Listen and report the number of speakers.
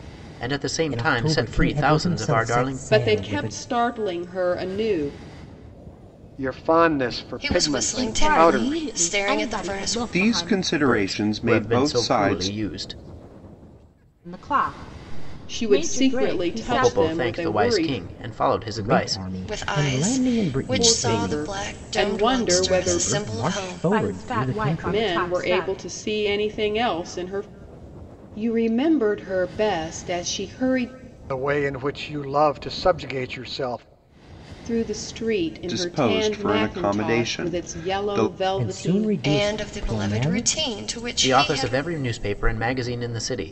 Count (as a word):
seven